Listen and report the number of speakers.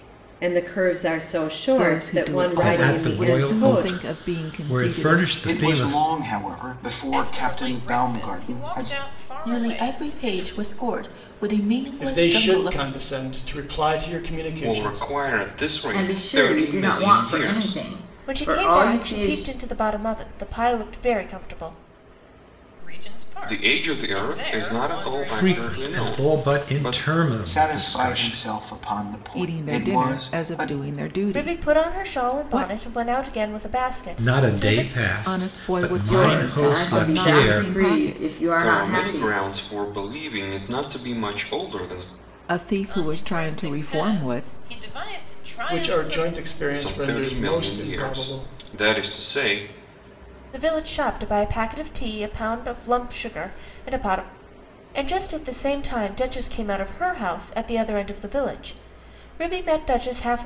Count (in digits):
10